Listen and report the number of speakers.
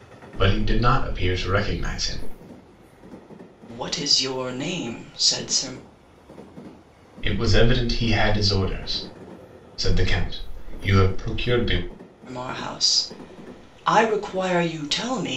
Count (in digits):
2